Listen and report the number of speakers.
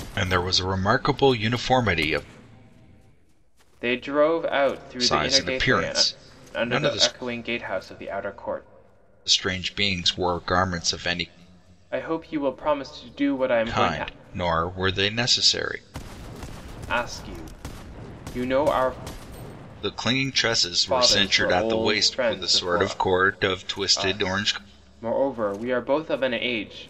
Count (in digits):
2